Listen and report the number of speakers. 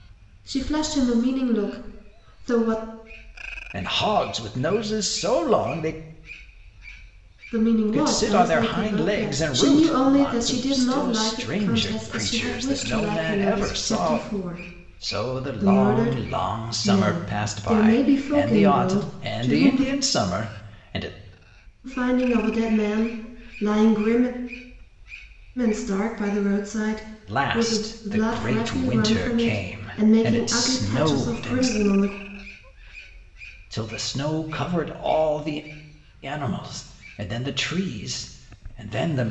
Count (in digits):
2